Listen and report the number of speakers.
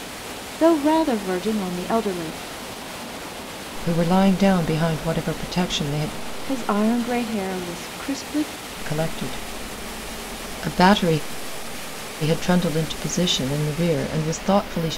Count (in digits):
2